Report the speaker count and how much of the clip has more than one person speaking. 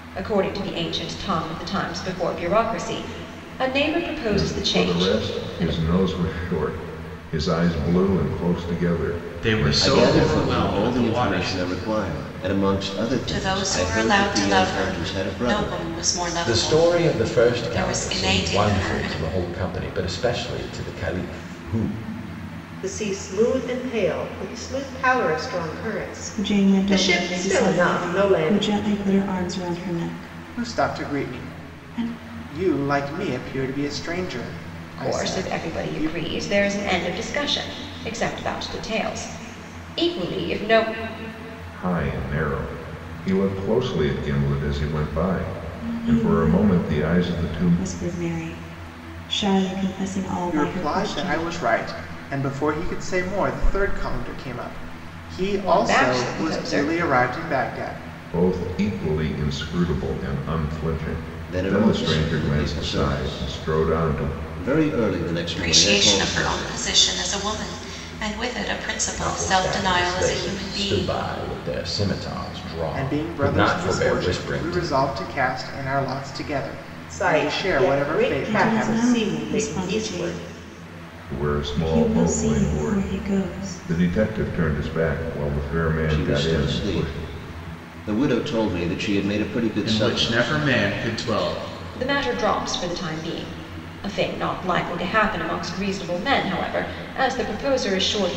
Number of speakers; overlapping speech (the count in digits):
9, about 36%